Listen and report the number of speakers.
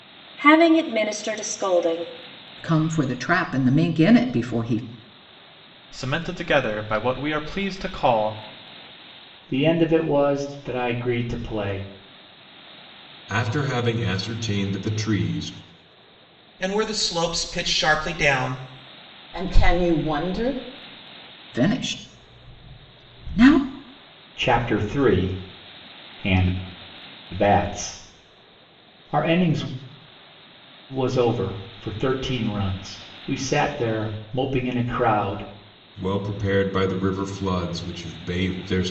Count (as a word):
seven